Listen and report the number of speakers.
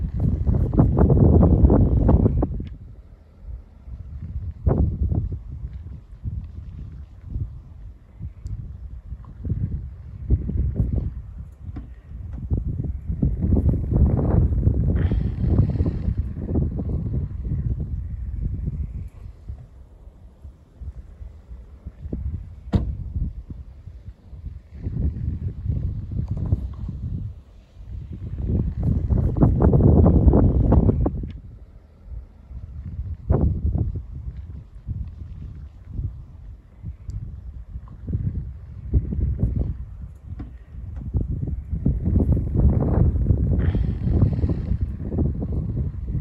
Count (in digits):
0